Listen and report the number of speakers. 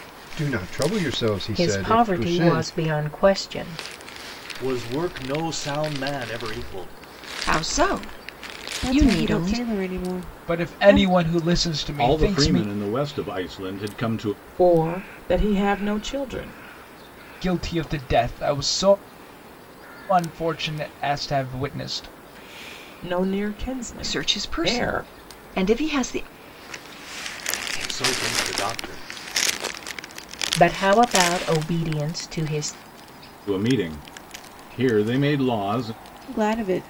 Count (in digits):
8